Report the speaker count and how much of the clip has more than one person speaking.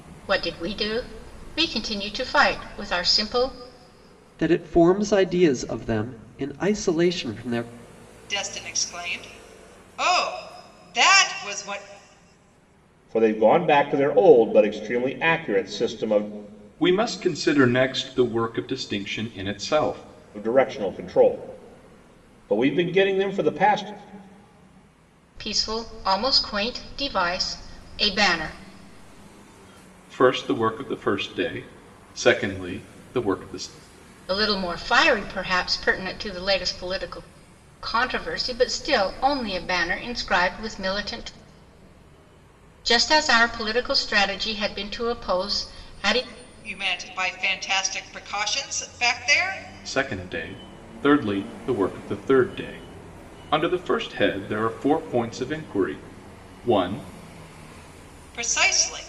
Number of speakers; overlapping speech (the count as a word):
five, no overlap